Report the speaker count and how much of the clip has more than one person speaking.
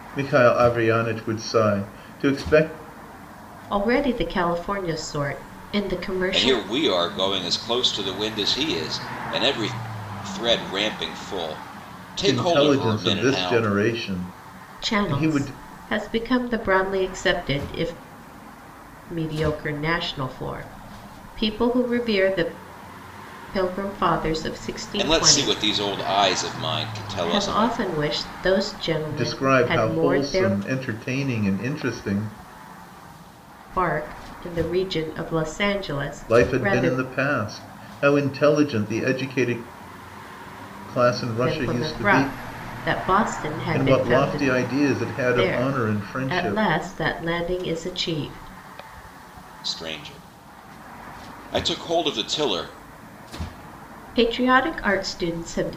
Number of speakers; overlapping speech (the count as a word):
three, about 16%